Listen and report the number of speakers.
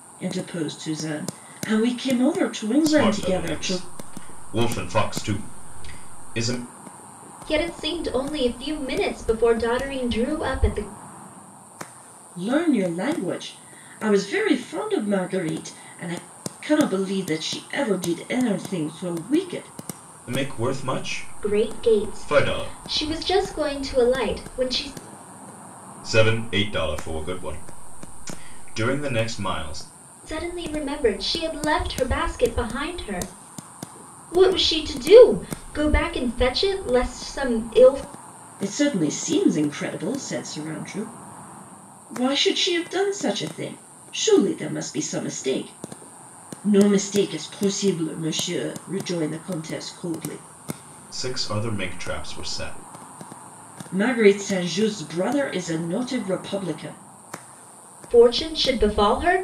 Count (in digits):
3